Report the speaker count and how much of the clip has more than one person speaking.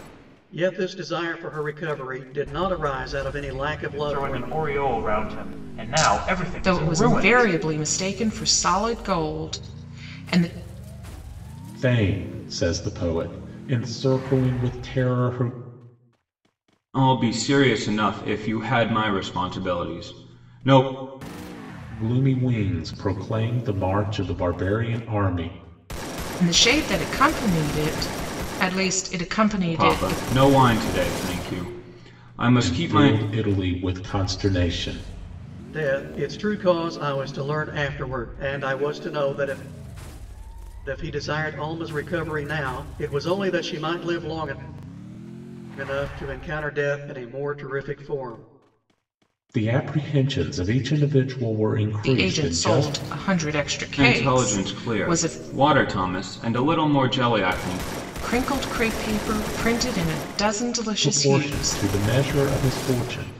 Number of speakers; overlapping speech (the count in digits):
5, about 9%